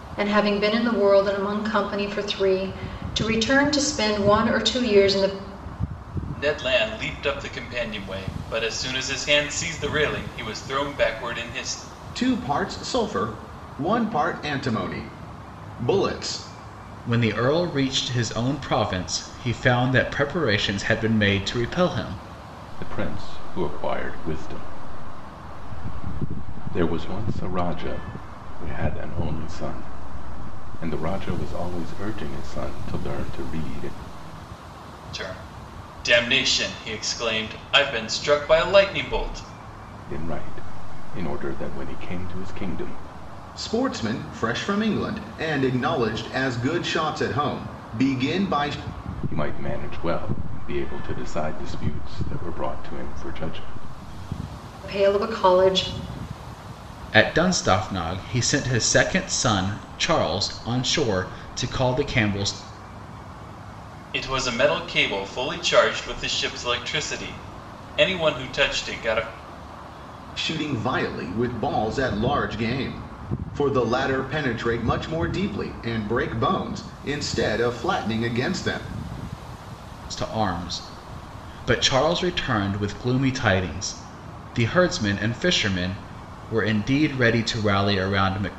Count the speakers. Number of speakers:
five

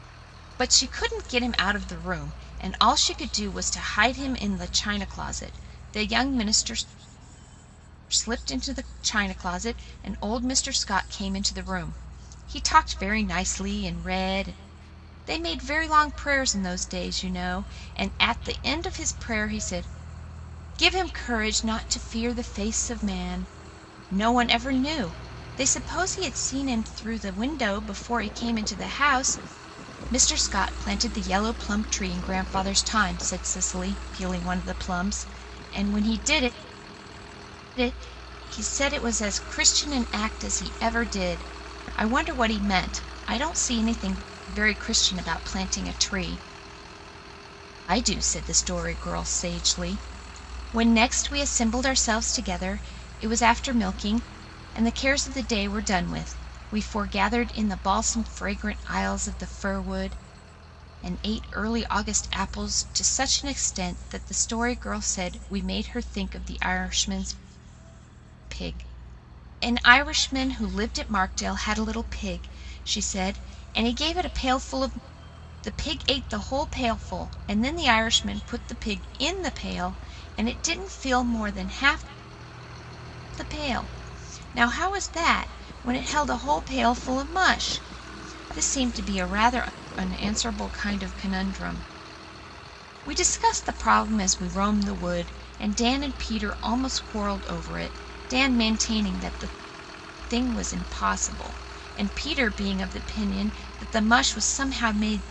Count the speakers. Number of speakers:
one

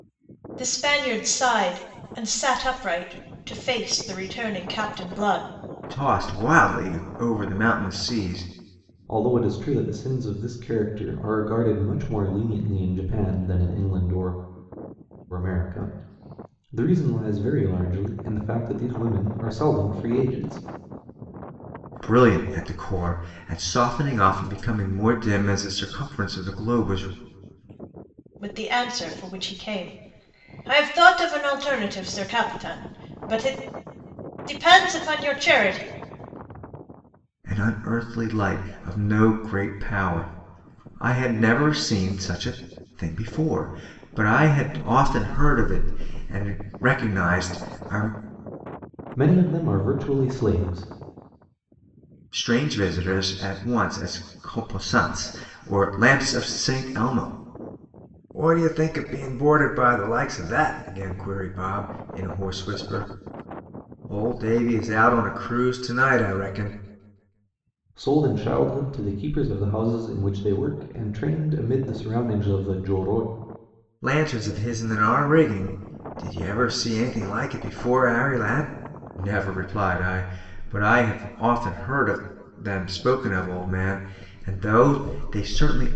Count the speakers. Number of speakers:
three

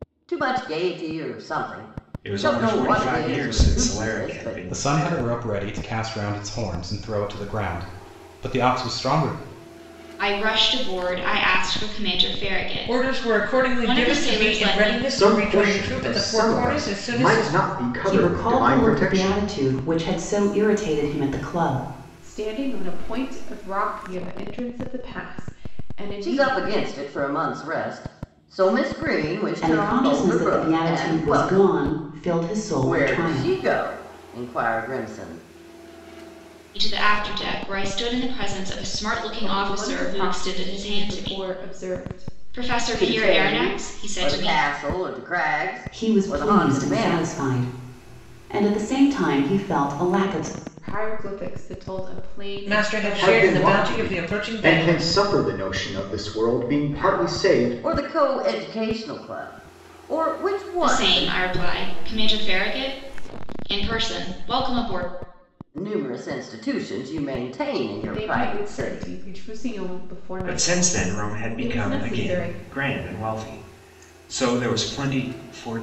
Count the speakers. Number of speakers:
eight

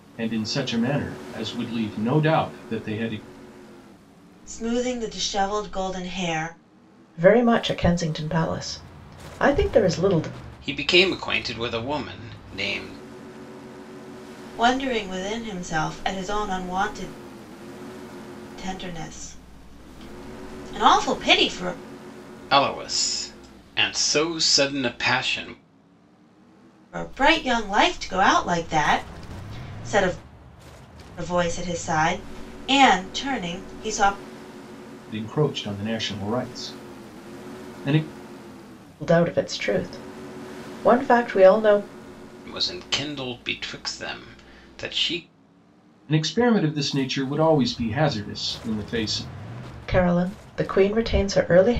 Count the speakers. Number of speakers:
four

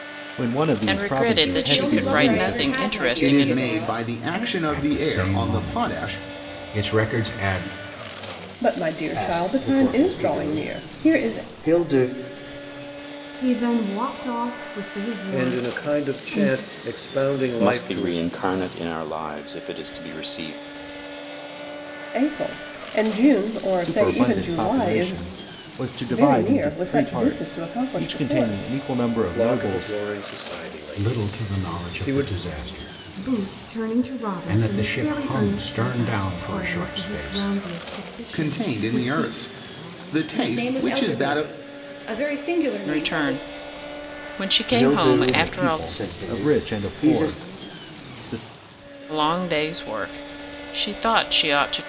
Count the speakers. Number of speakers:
ten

